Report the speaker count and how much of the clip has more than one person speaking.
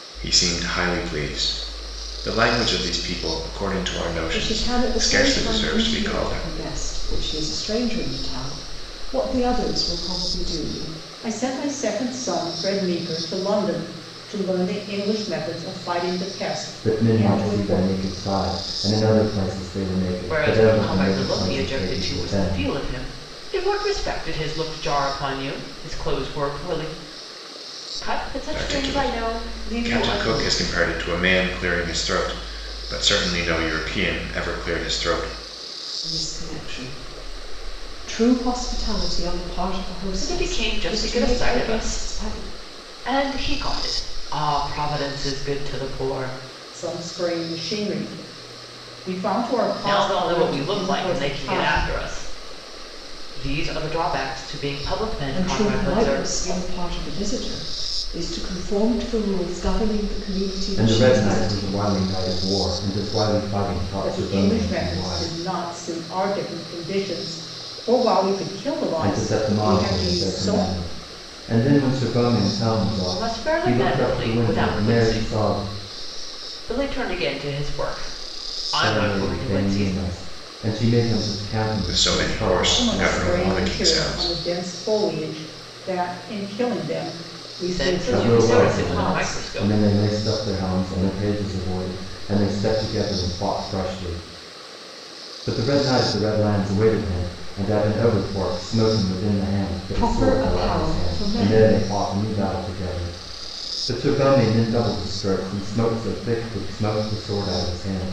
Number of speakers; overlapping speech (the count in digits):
5, about 26%